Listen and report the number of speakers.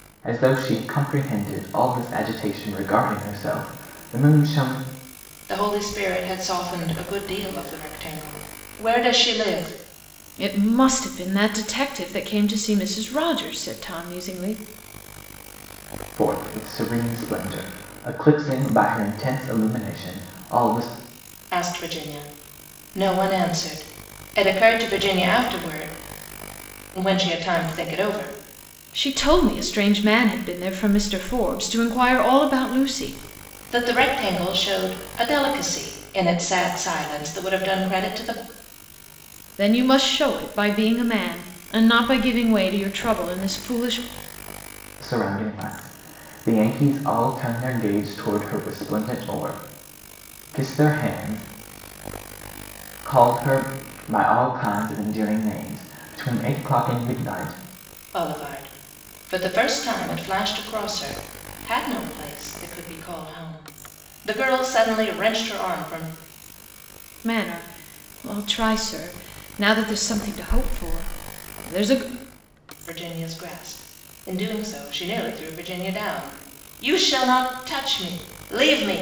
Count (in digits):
3